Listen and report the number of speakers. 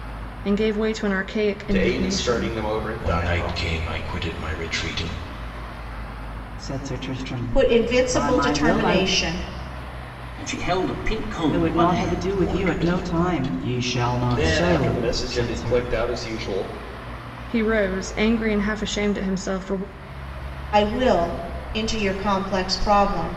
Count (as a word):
six